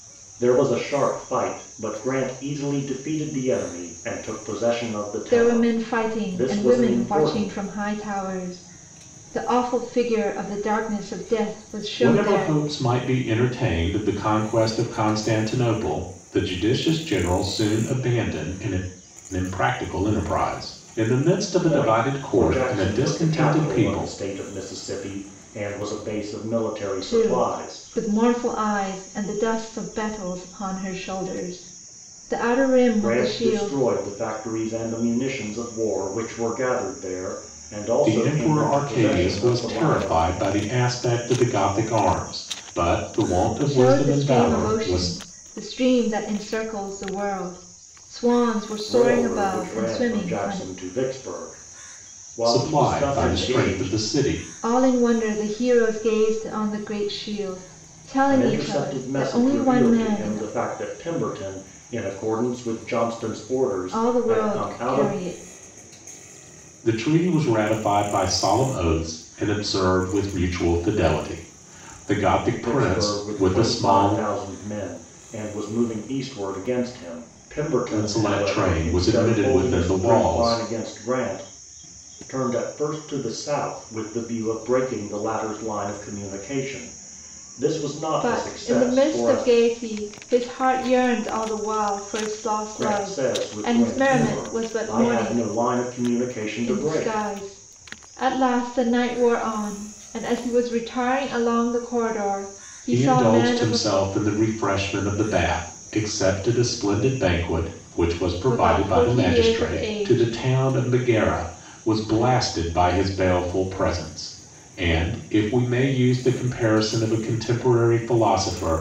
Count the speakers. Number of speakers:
three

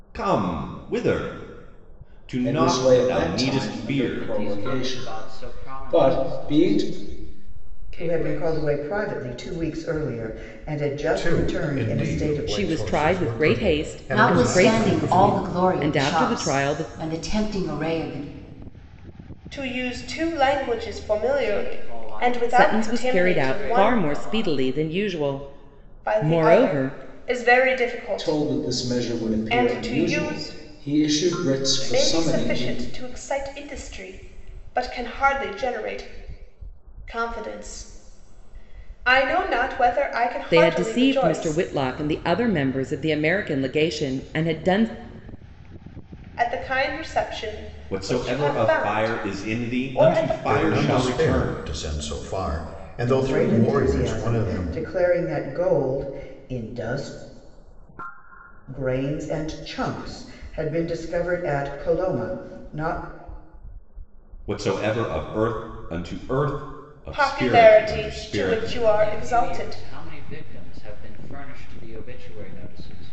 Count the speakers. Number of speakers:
eight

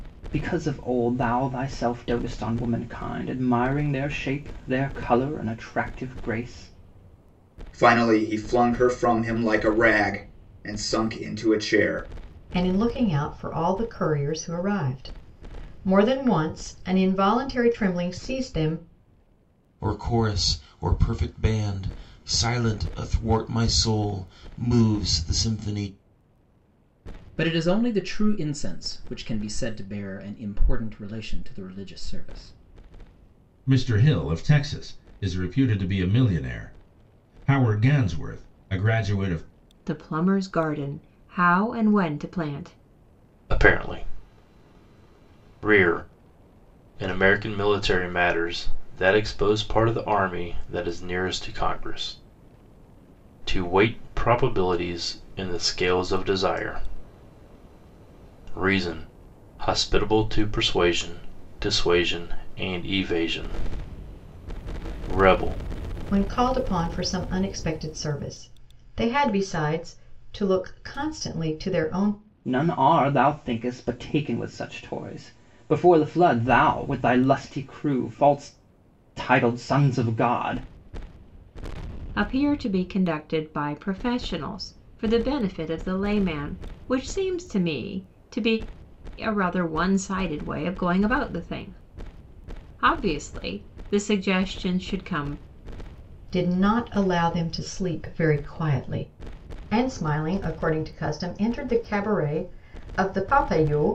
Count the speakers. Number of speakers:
eight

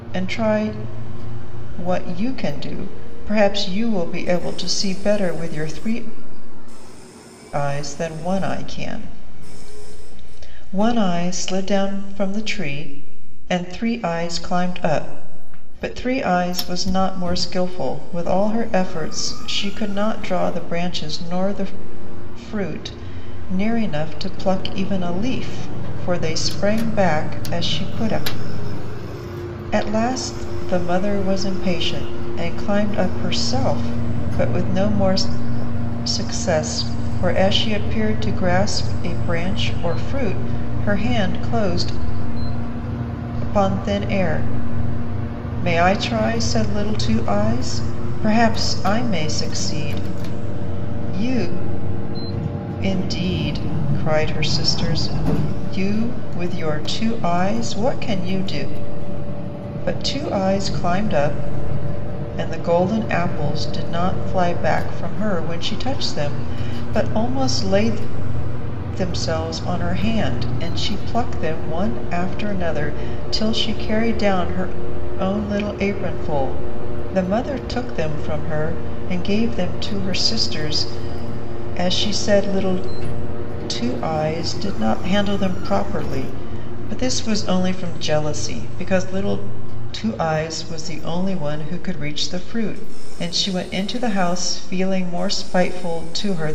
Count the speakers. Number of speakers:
one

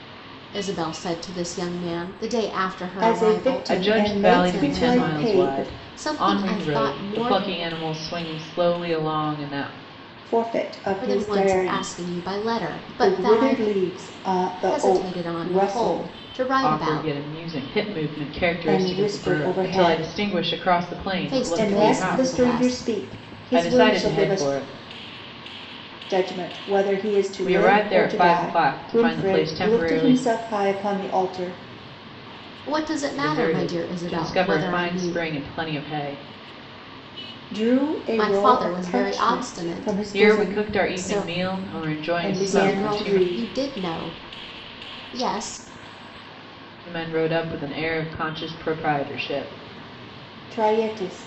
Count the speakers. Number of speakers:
three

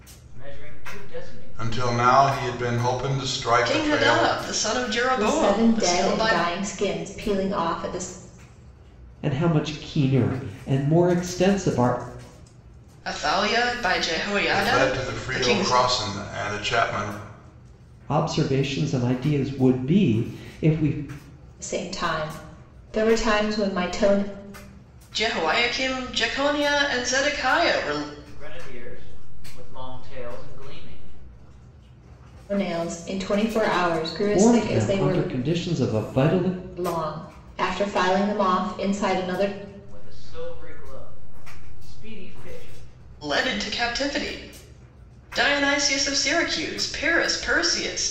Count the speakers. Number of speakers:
five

